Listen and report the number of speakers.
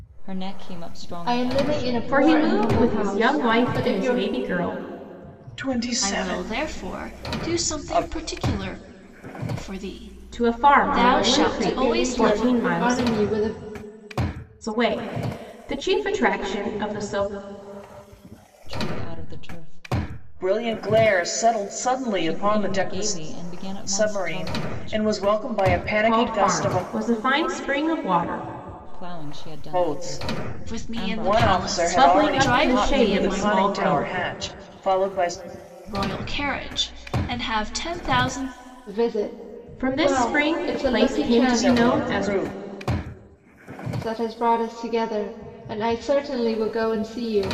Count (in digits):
5